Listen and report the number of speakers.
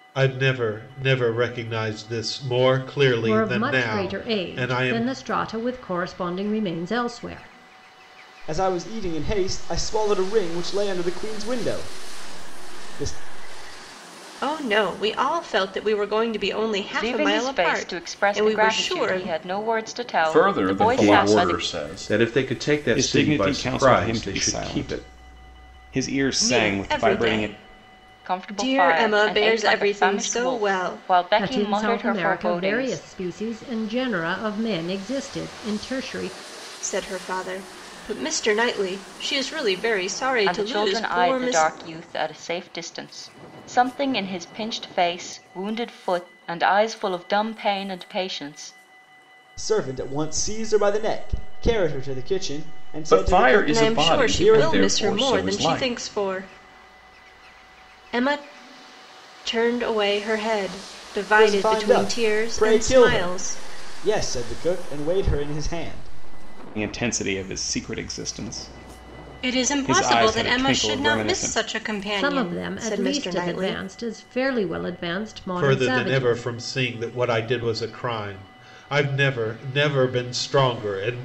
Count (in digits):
8